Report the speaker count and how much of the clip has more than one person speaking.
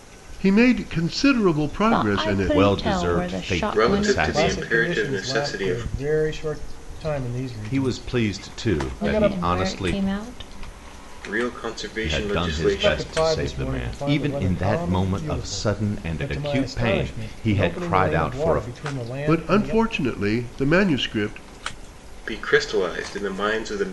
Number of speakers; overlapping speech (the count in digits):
5, about 57%